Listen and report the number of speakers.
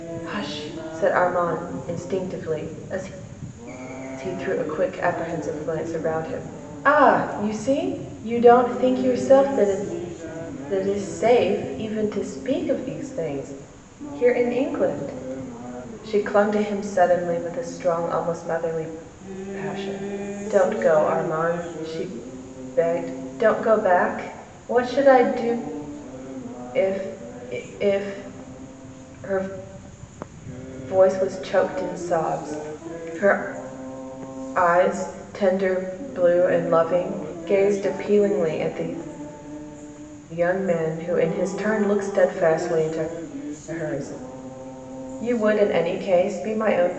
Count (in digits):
1